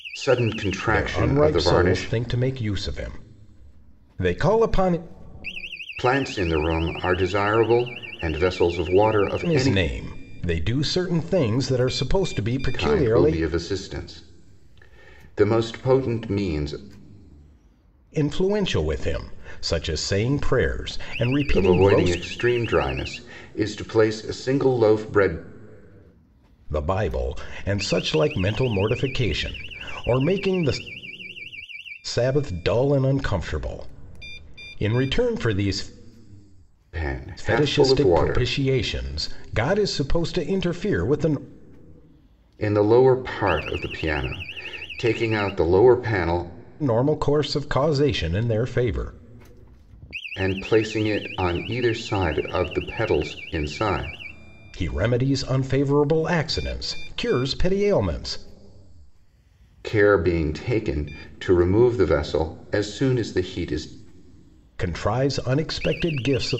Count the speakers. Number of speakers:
two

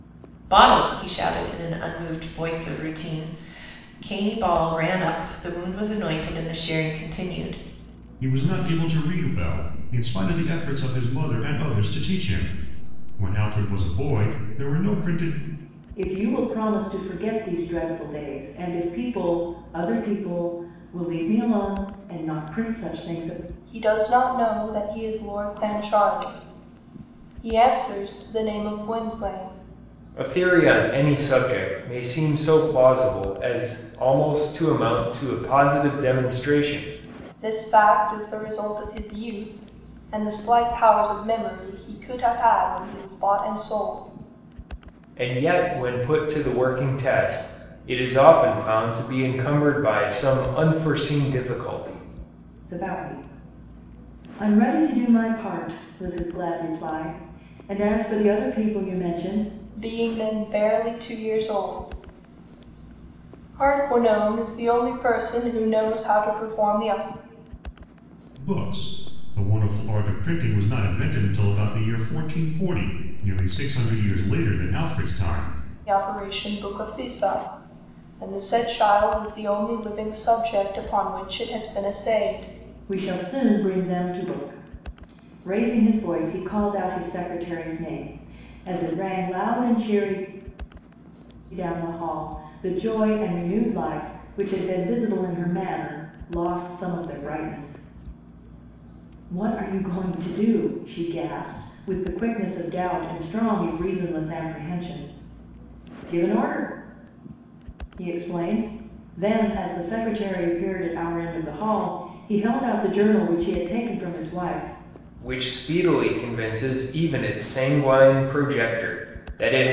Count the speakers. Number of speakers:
five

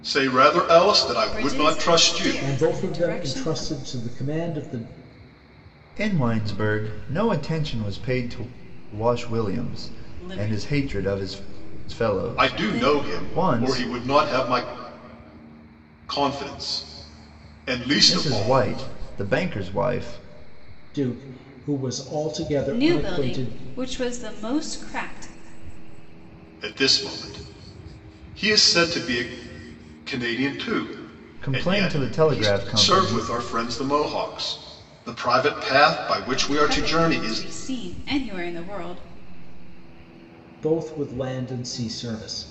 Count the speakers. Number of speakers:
four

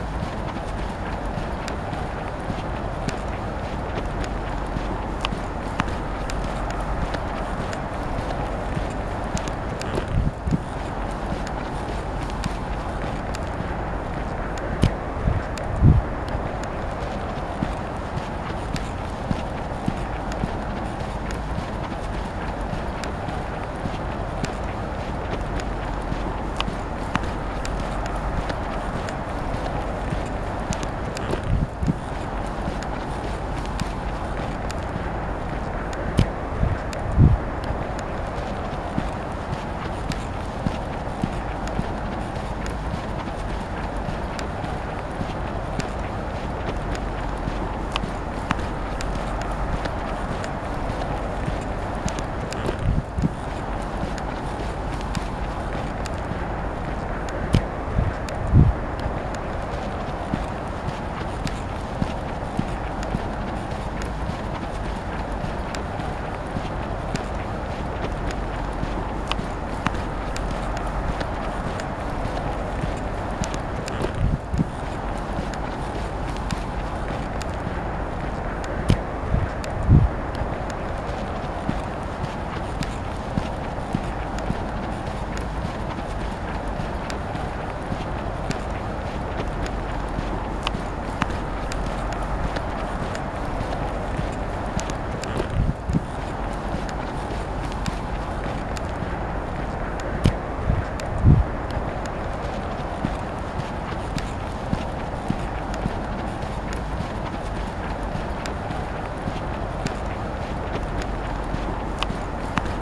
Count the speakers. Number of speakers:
zero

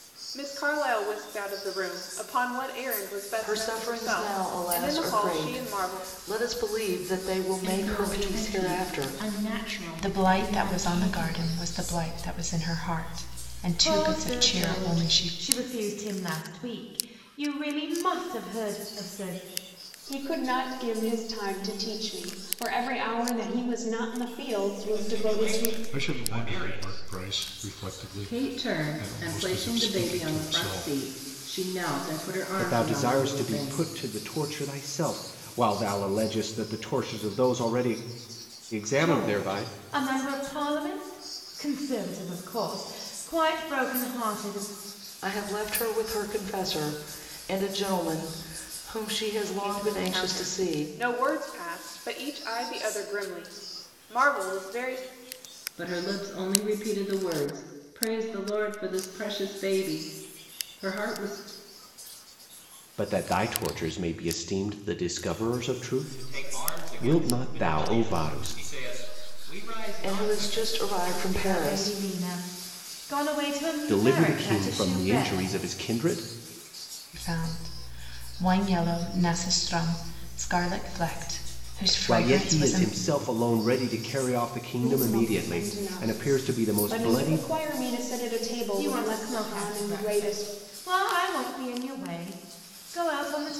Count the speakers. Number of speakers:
ten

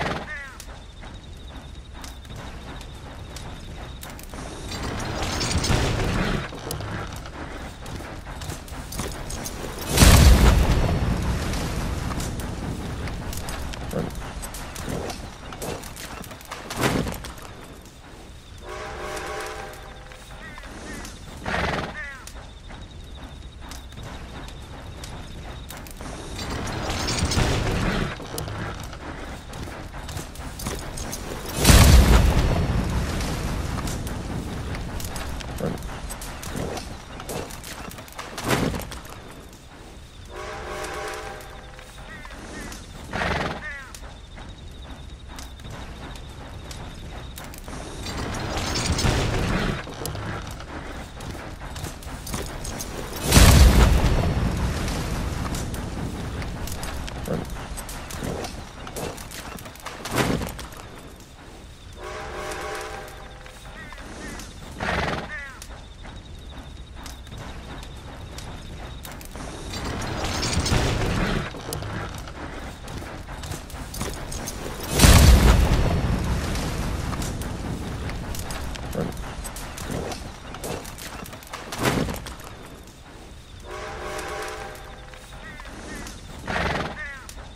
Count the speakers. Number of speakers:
zero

